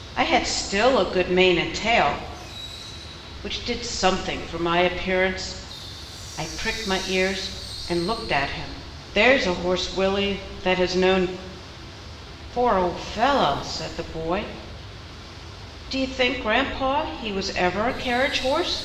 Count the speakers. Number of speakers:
1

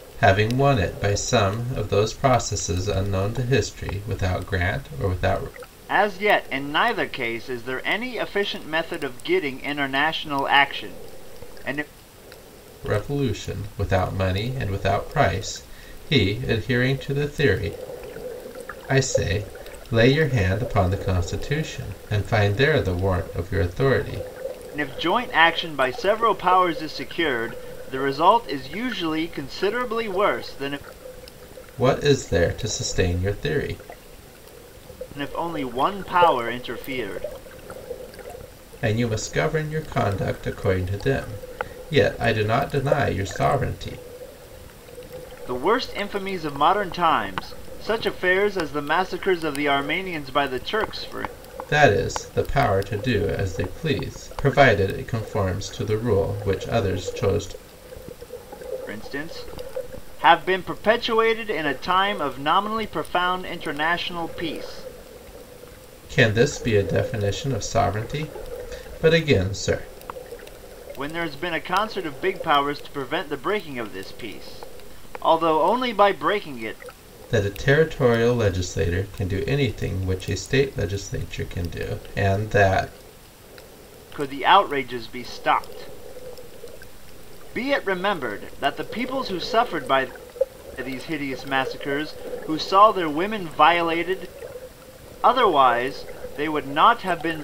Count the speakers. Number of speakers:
2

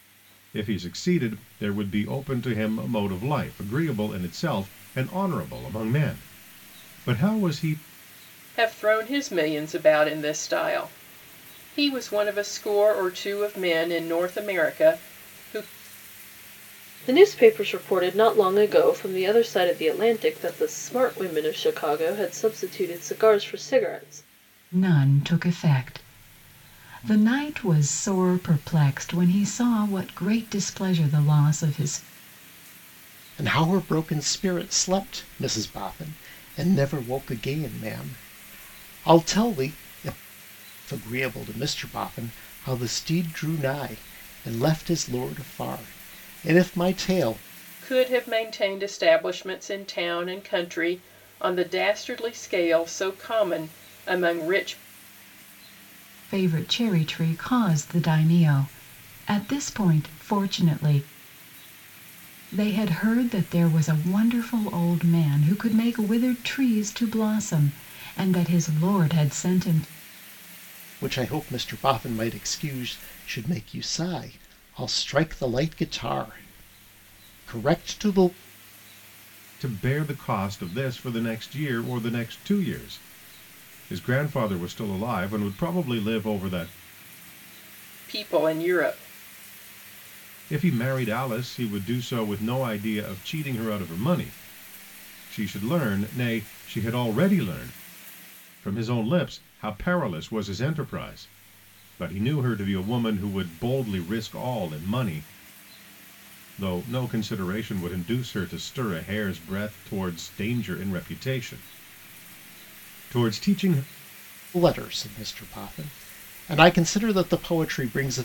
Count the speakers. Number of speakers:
5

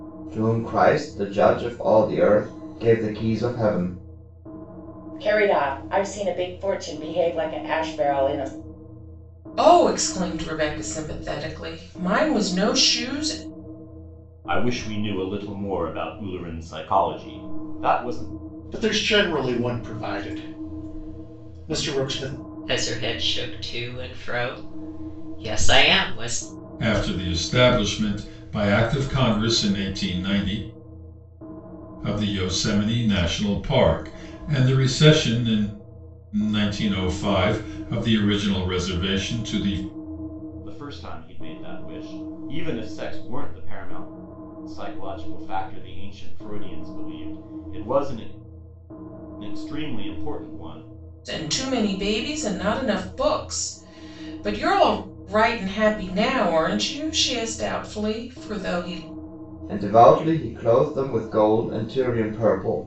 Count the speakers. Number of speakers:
7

